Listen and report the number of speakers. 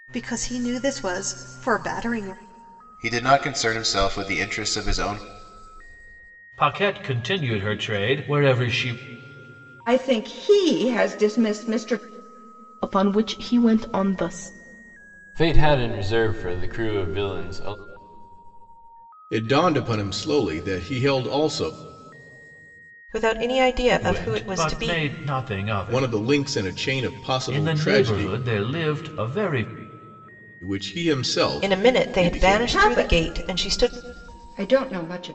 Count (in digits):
8